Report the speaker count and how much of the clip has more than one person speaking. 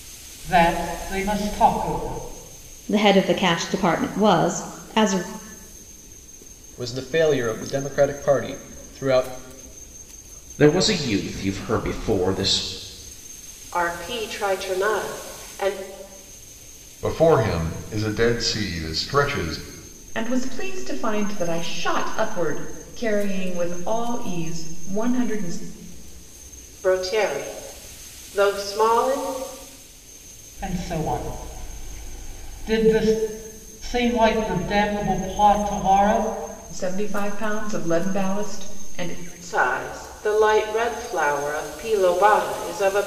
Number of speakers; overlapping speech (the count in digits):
7, no overlap